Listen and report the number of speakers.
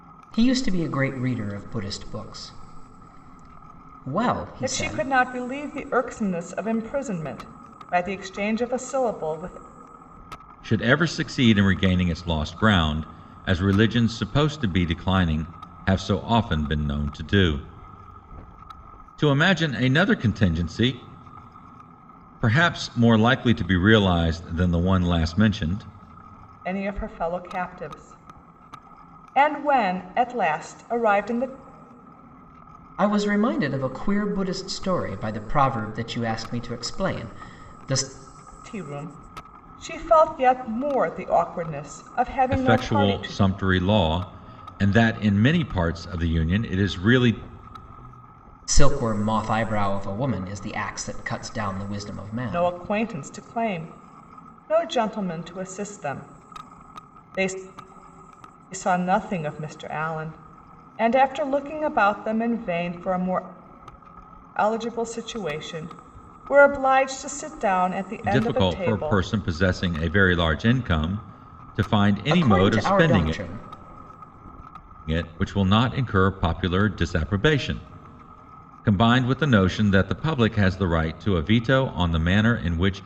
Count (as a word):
three